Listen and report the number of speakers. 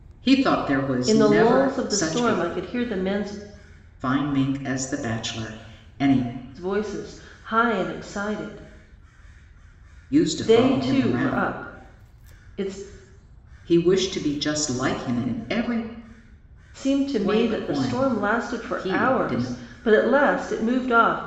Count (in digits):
2